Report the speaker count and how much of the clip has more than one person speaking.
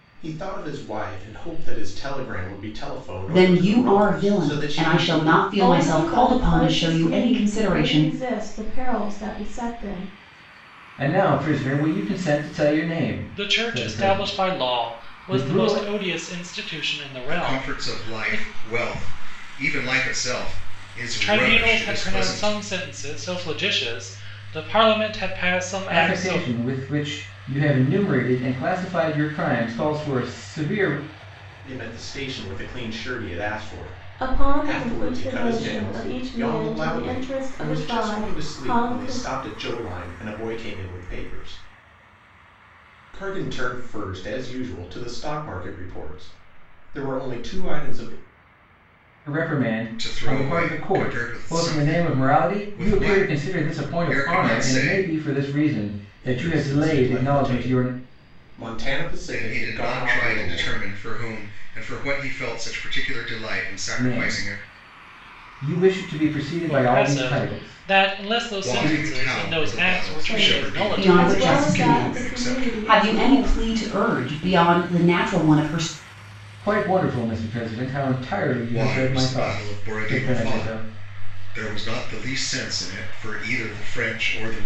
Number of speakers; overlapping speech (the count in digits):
6, about 39%